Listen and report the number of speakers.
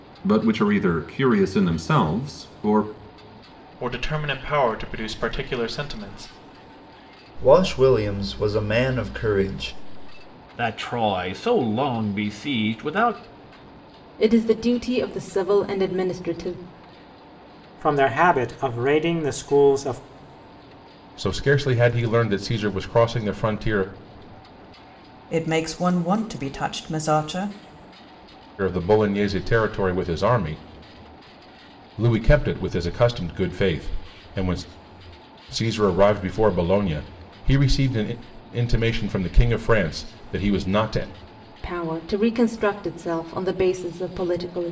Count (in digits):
8